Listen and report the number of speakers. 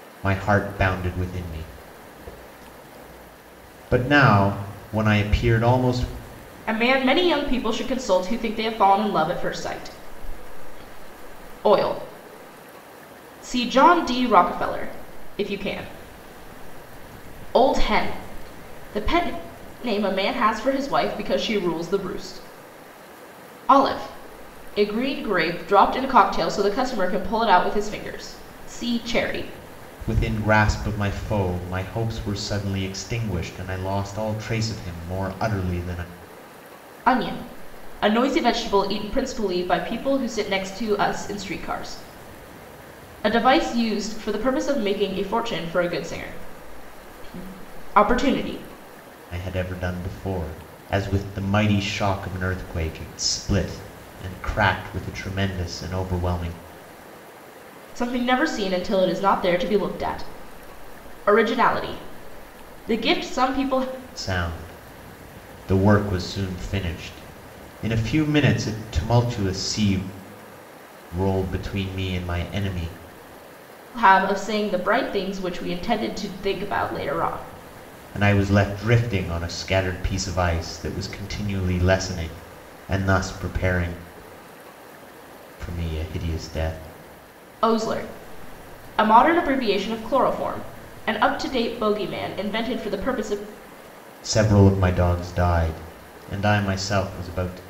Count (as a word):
two